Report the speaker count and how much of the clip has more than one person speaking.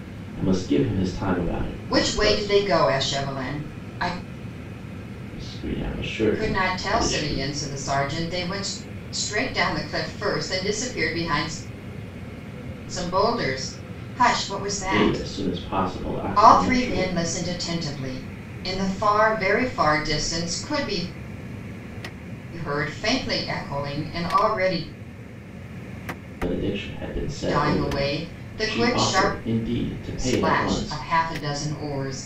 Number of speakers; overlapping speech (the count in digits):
2, about 17%